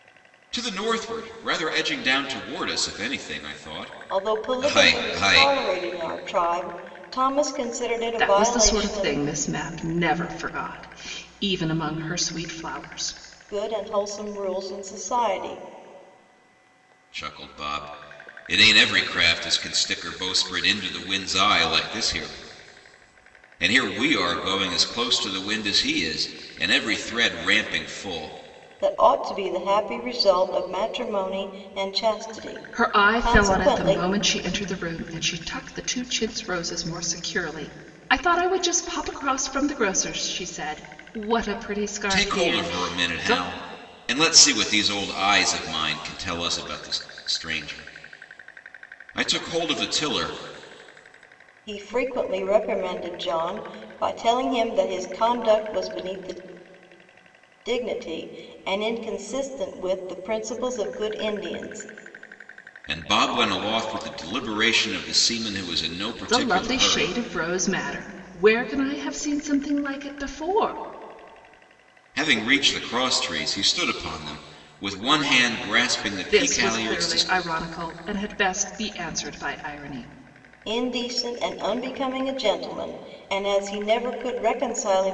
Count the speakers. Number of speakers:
three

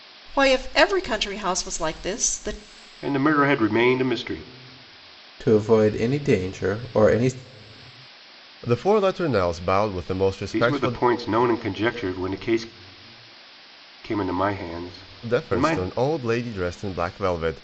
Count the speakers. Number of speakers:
four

